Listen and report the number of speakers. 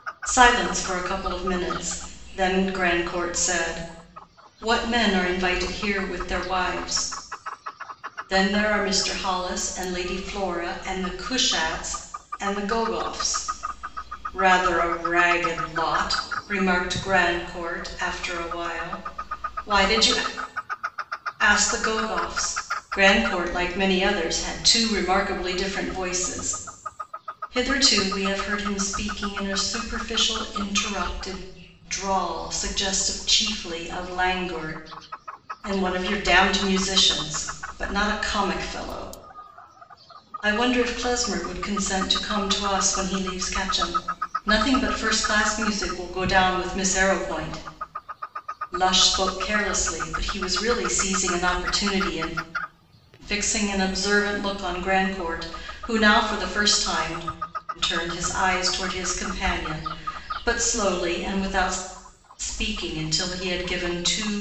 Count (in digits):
1